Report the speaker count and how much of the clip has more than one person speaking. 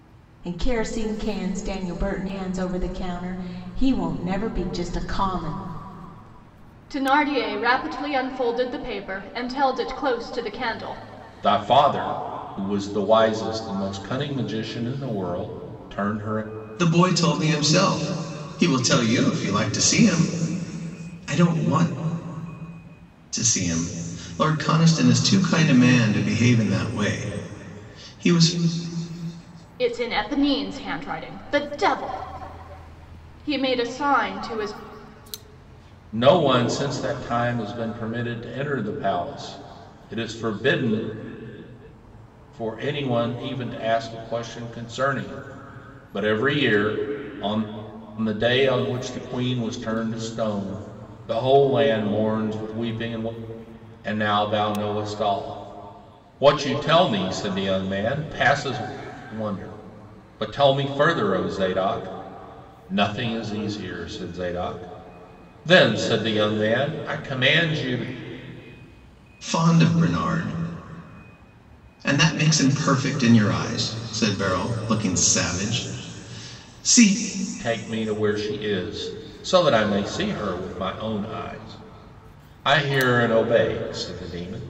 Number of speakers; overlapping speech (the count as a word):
four, no overlap